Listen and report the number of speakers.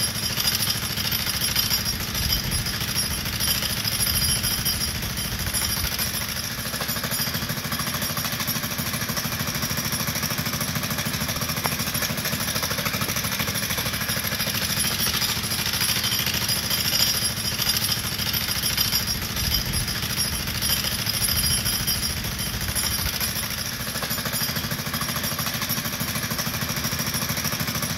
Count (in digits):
0